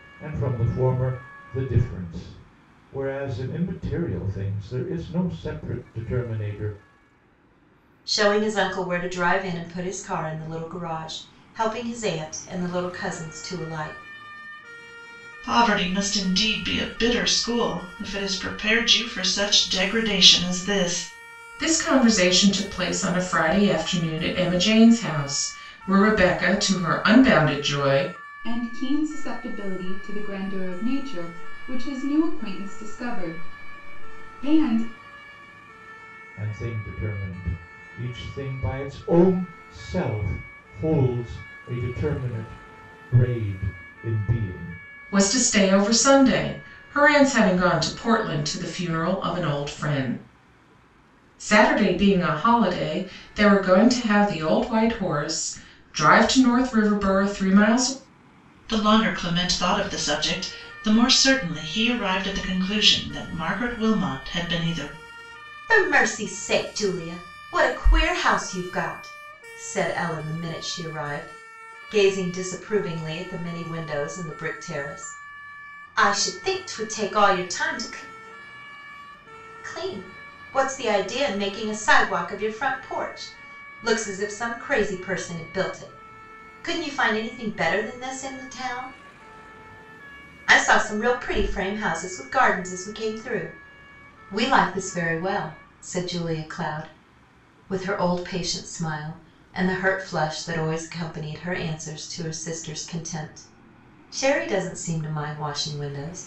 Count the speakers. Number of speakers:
5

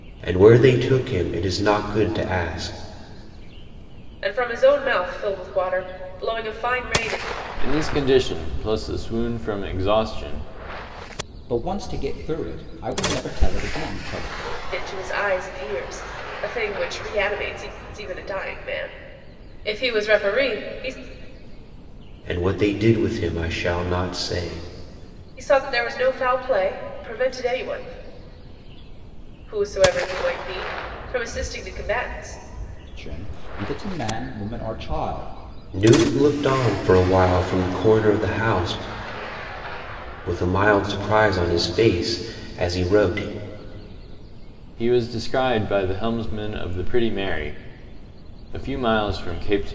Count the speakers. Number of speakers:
4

